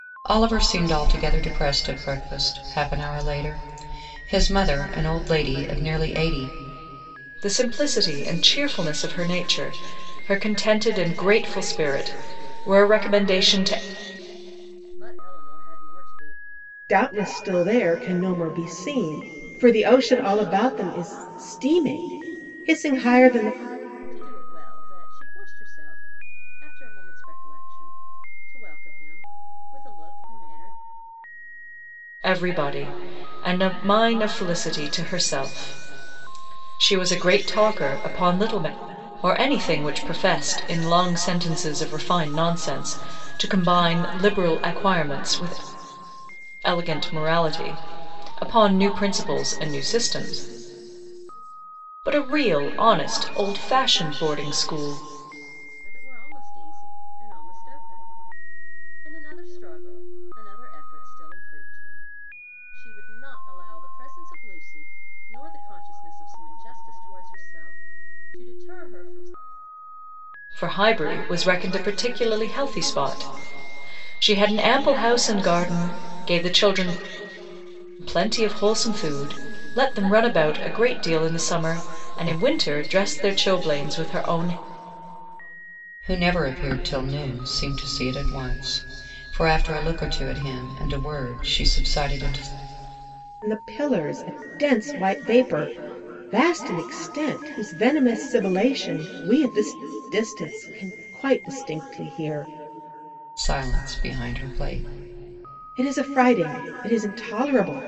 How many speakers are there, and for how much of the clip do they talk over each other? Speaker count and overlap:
4, no overlap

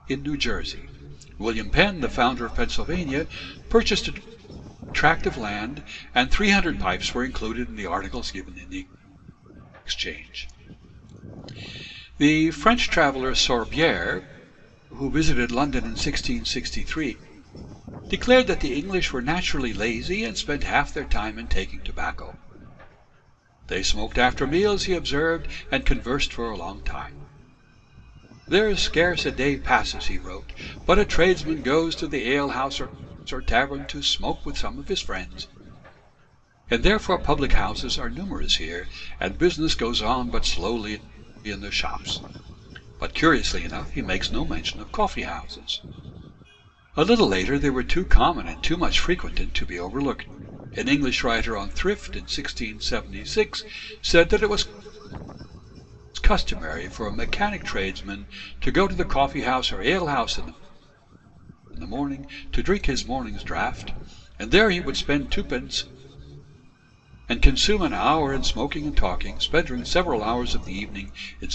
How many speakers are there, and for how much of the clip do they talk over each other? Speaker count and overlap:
1, no overlap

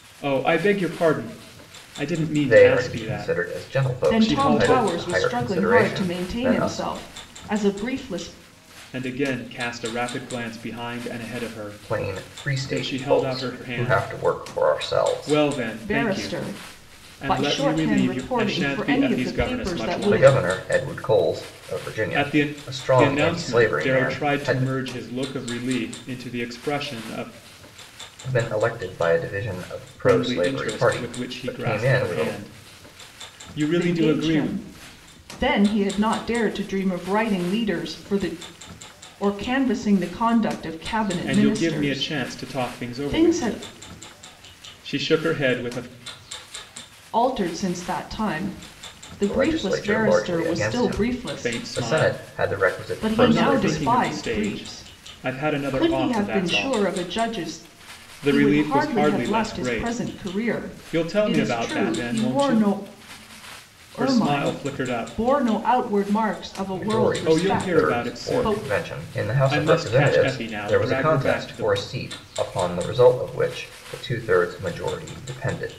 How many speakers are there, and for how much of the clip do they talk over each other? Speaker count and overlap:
3, about 53%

